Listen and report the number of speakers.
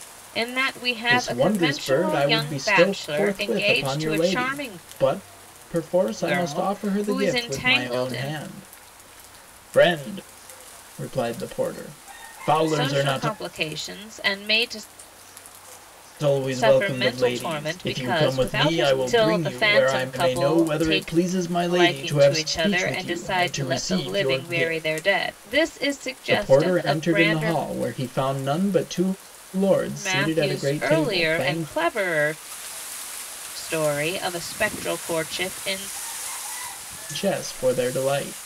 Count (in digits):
2